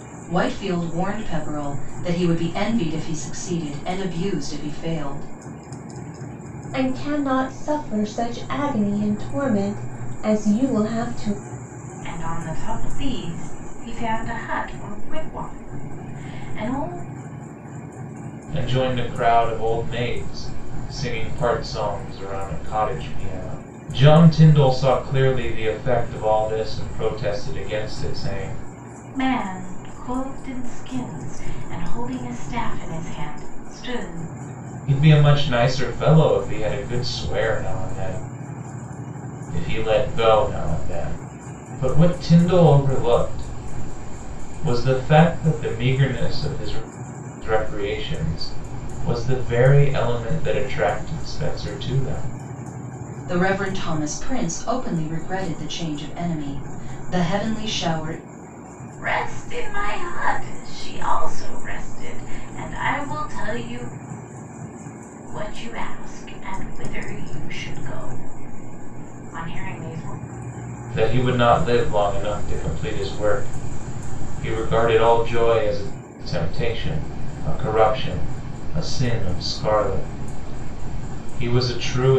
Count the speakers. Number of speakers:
4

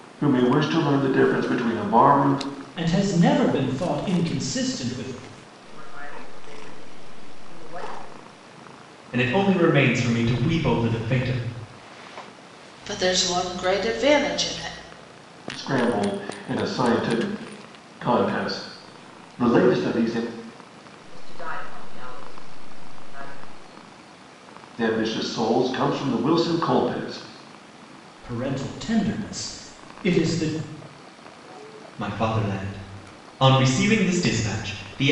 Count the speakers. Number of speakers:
5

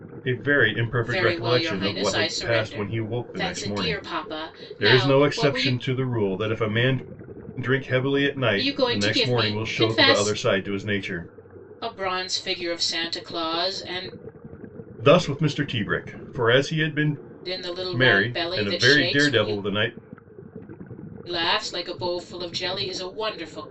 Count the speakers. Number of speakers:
2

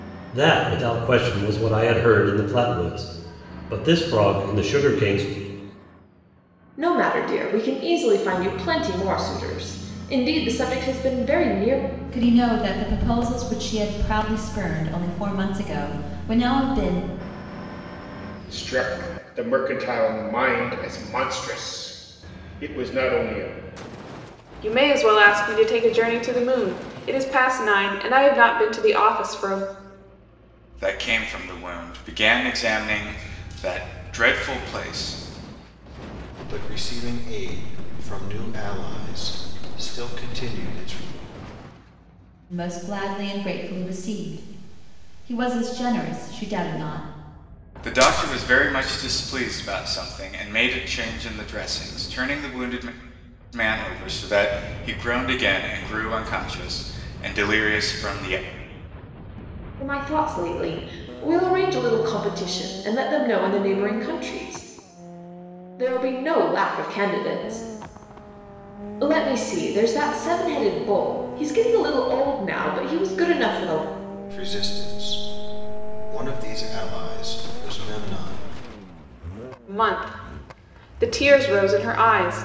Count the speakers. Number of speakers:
7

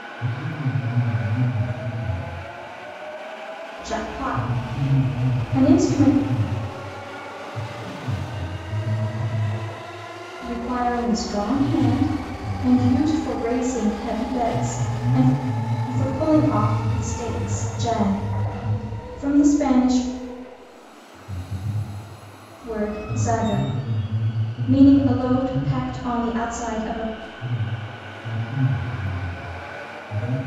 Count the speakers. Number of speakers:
2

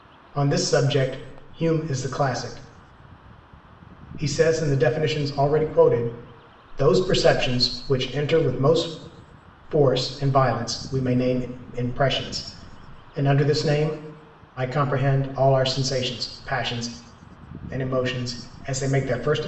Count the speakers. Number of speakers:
1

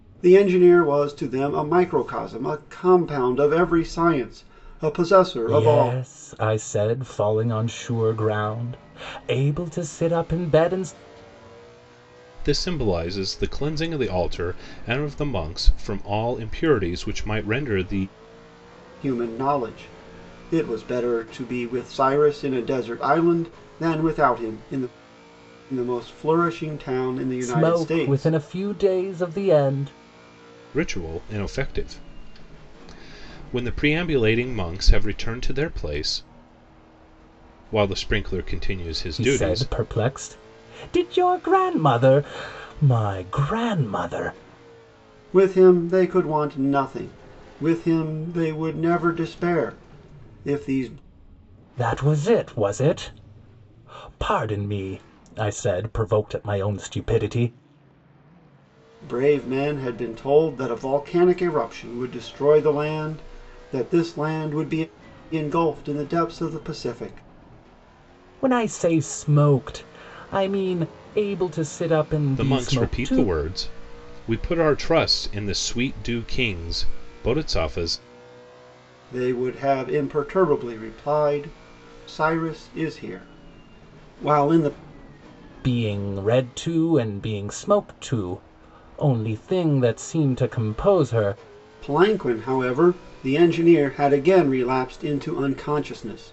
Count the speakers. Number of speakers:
3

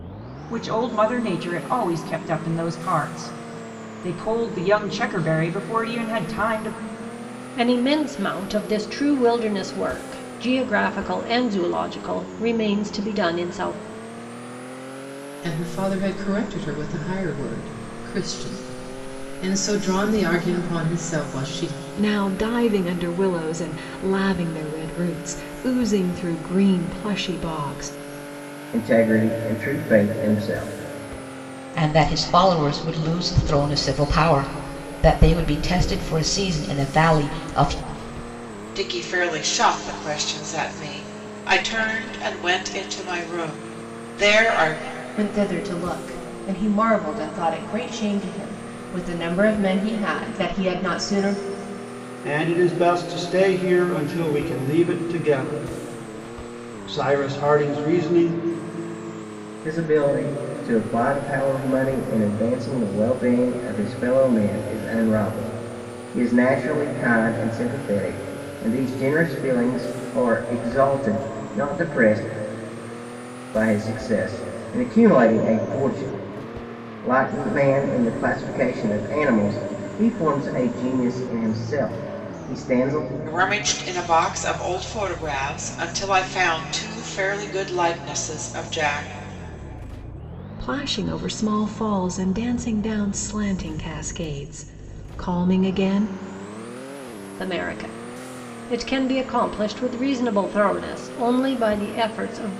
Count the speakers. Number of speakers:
9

